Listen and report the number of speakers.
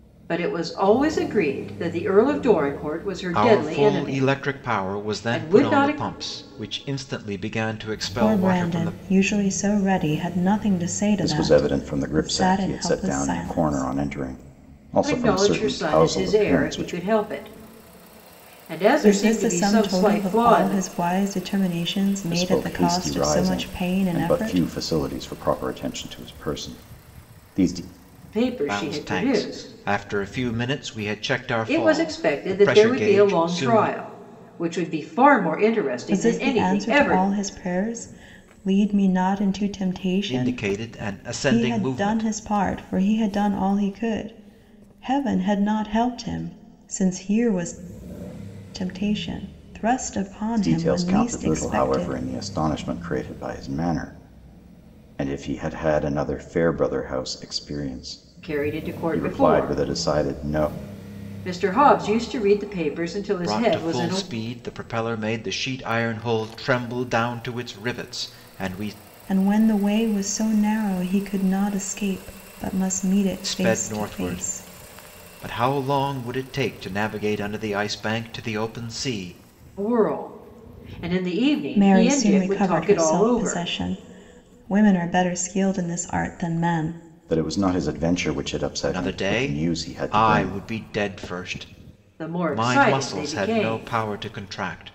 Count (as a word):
four